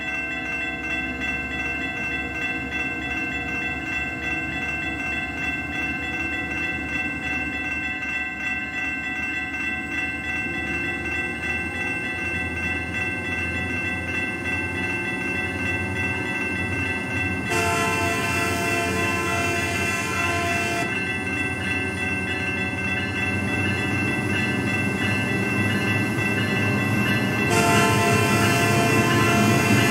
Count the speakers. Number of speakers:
0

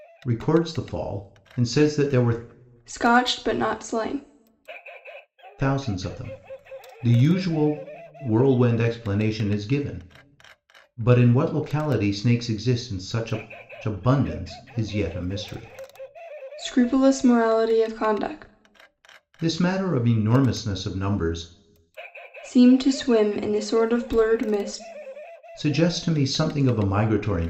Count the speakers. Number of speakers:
2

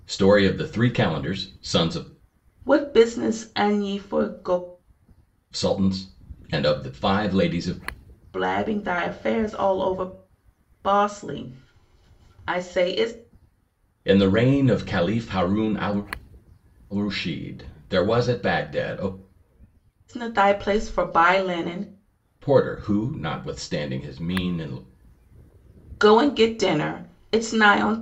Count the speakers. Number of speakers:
2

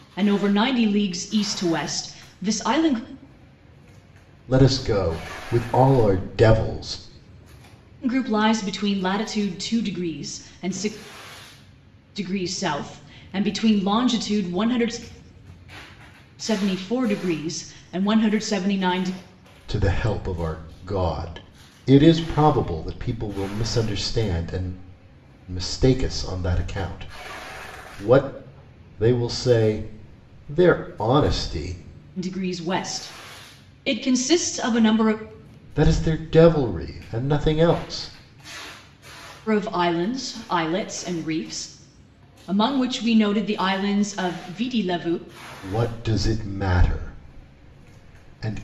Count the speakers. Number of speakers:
2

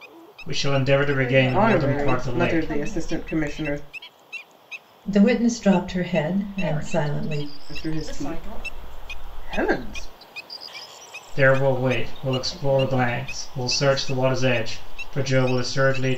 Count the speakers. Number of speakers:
4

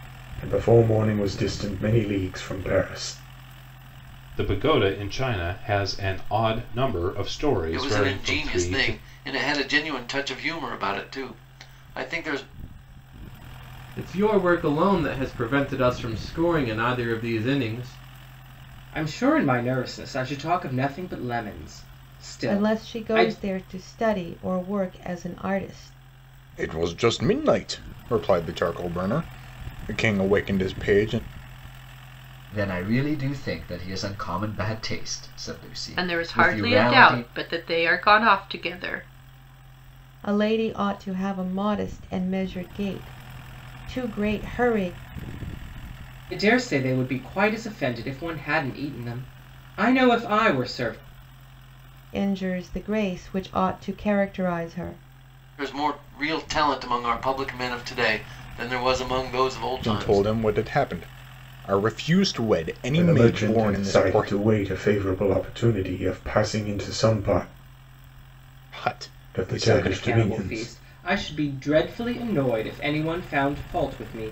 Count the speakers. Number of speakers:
9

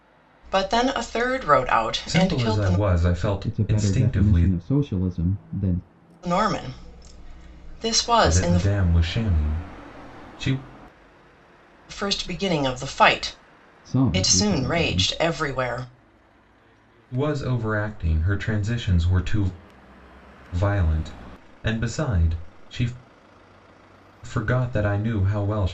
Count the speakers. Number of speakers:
3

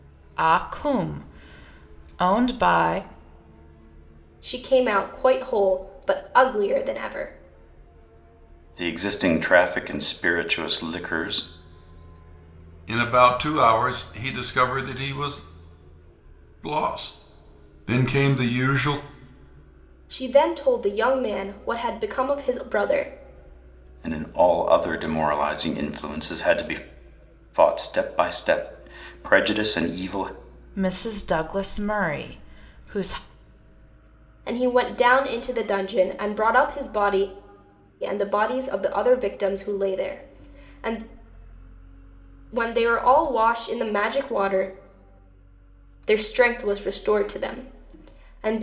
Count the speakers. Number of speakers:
4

